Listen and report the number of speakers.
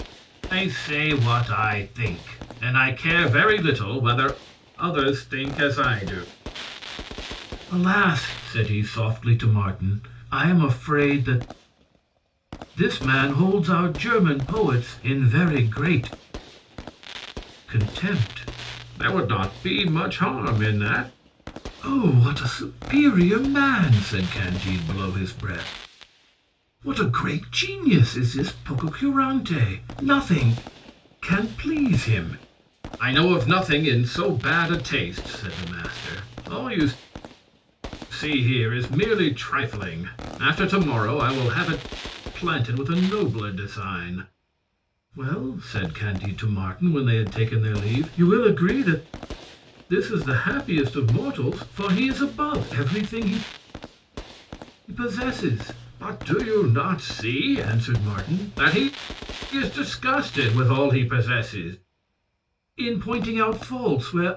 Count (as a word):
one